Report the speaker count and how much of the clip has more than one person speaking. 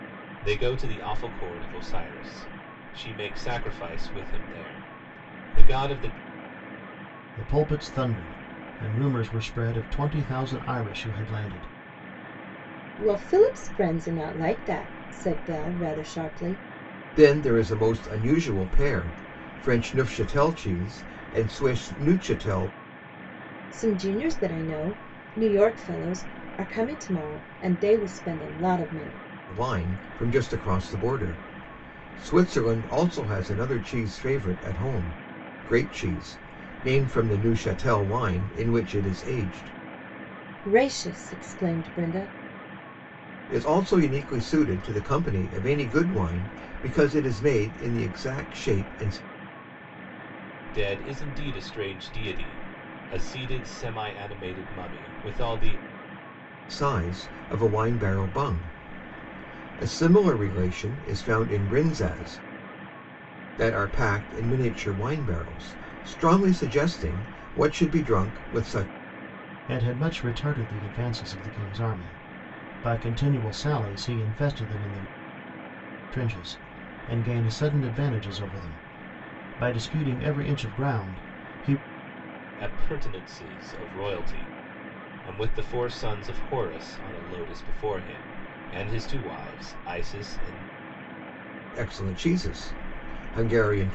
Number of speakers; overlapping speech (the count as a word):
four, no overlap